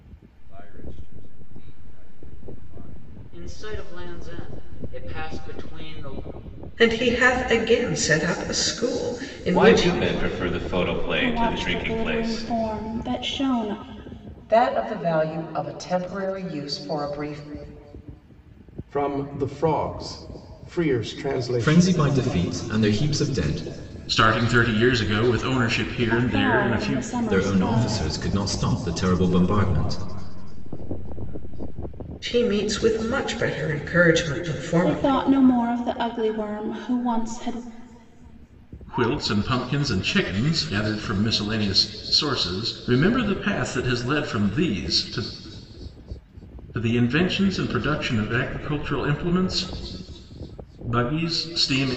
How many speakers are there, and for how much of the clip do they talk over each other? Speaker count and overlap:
9, about 10%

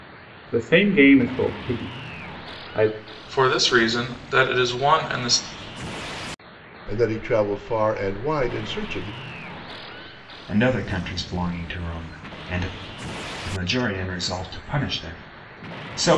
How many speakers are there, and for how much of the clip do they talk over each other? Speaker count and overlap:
4, no overlap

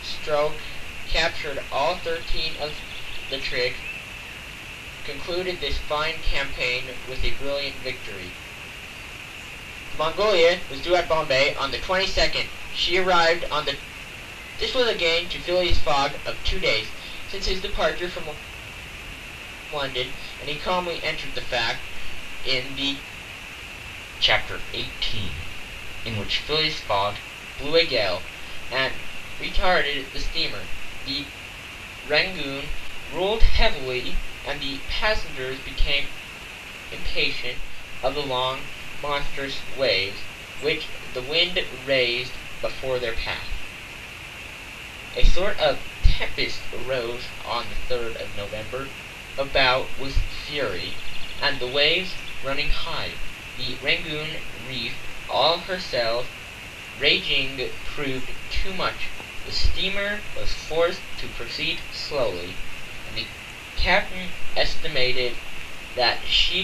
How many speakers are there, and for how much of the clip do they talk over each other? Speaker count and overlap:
1, no overlap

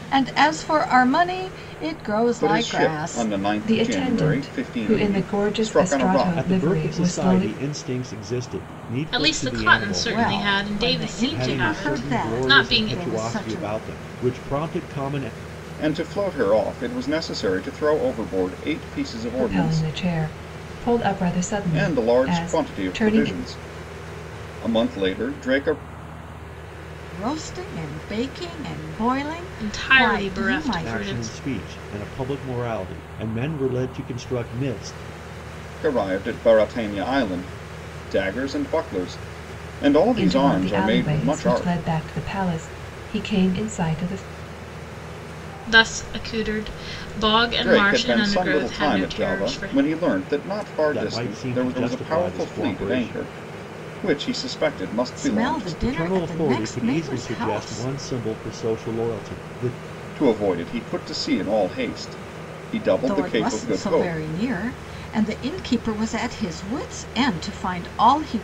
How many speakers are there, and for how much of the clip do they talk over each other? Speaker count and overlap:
5, about 35%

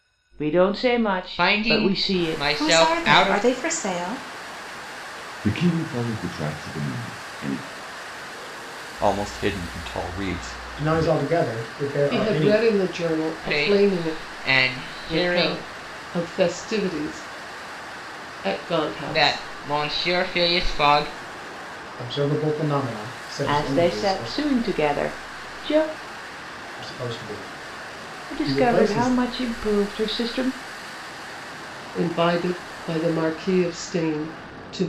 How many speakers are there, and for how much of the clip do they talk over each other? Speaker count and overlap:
7, about 19%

